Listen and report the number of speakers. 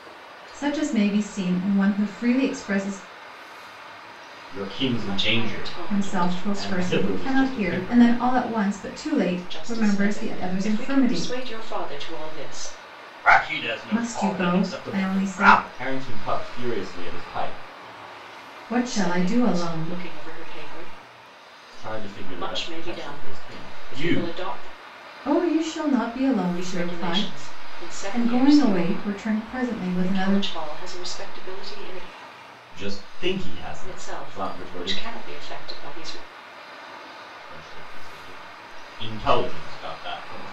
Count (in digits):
3